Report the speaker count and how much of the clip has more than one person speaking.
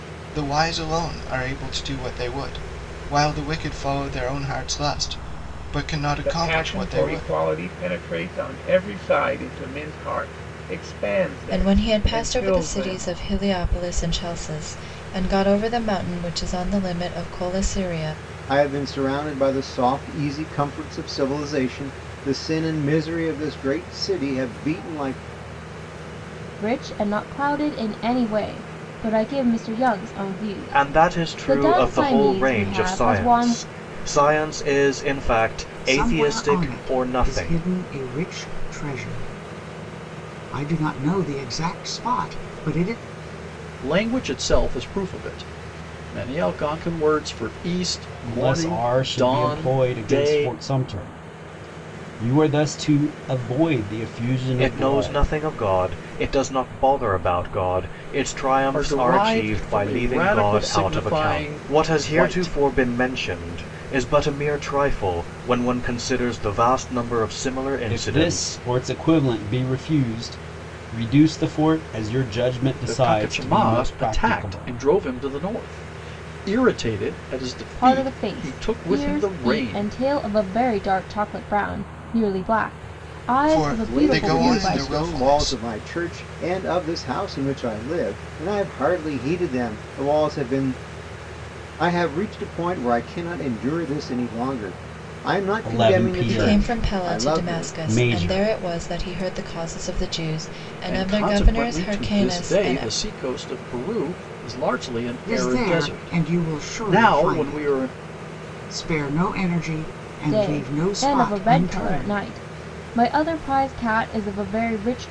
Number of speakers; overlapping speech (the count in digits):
9, about 27%